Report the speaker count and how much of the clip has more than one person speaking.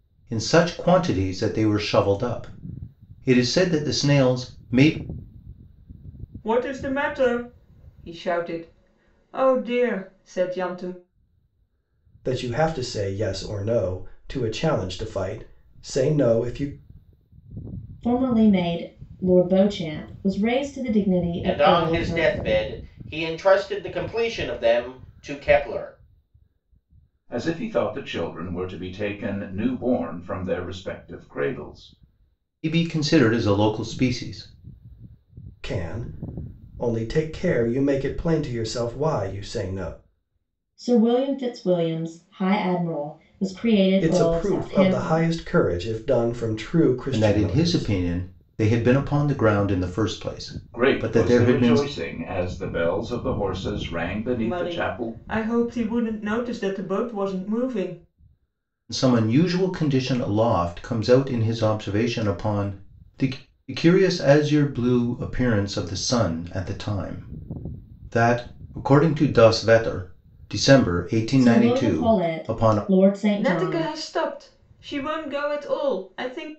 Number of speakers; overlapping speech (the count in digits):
6, about 9%